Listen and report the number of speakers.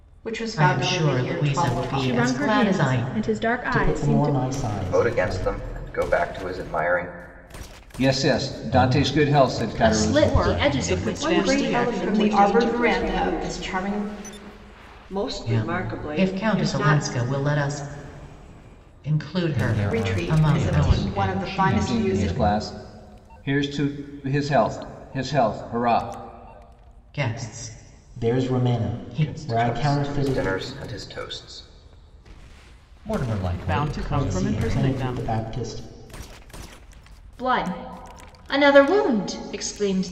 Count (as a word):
ten